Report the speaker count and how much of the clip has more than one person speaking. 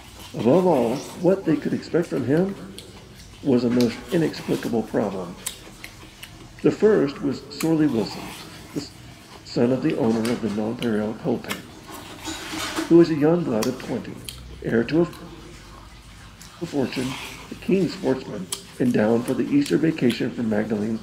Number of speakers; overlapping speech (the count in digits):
1, no overlap